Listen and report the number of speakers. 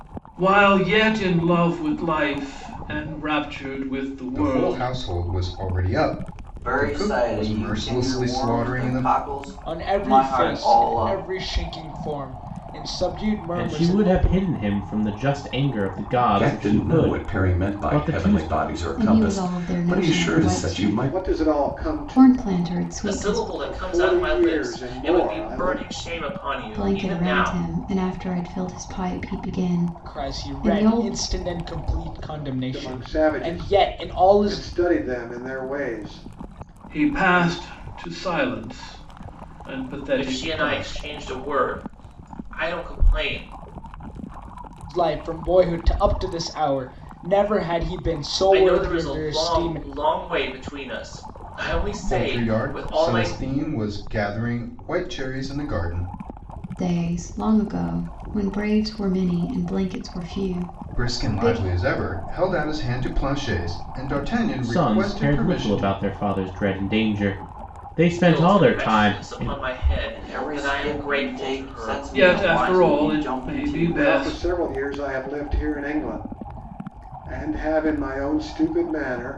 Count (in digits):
9